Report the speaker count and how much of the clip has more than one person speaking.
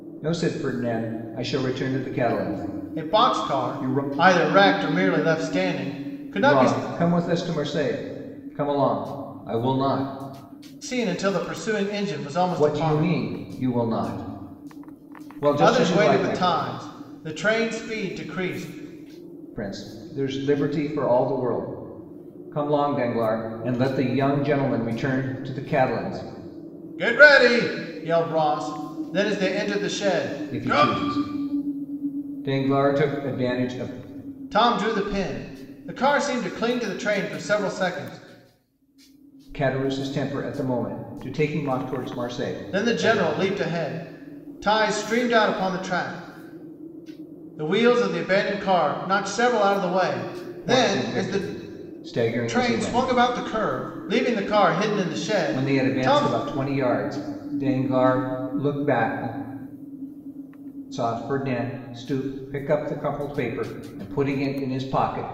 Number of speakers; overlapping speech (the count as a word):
two, about 10%